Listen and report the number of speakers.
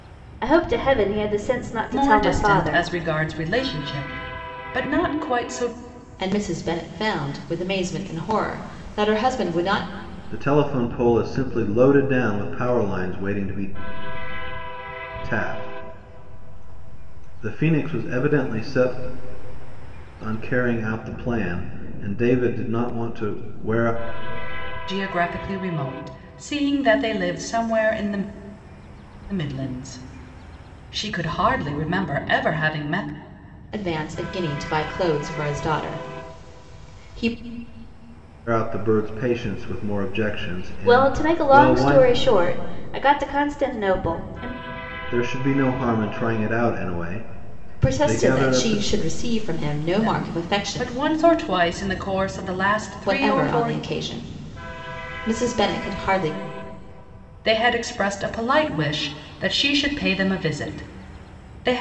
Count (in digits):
4